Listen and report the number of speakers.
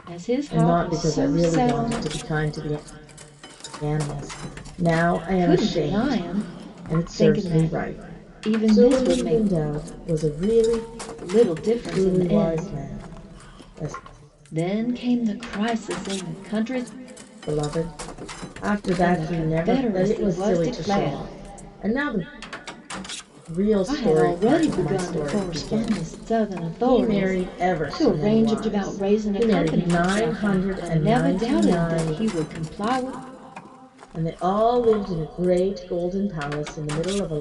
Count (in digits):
2